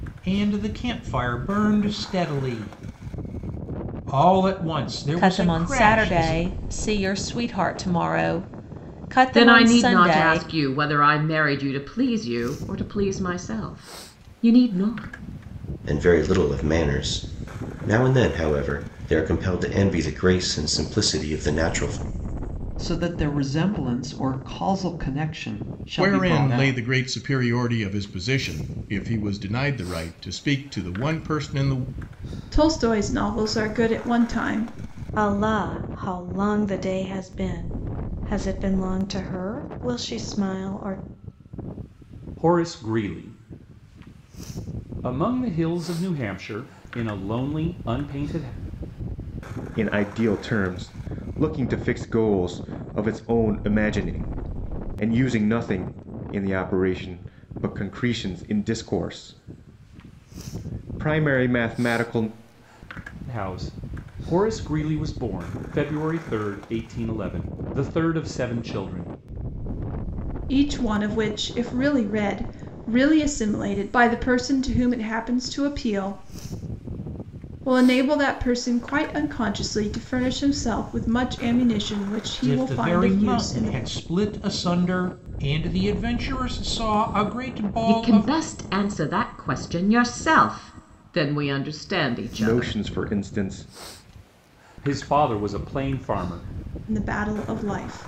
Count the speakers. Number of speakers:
ten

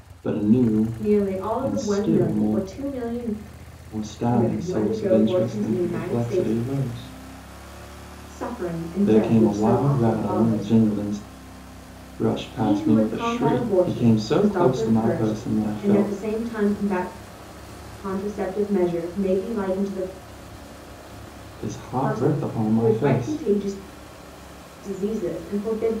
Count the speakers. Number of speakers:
two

